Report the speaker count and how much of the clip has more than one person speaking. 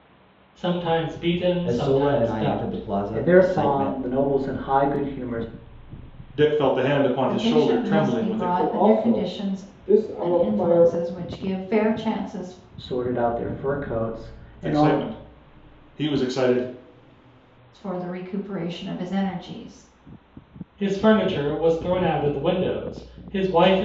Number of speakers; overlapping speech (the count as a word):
six, about 25%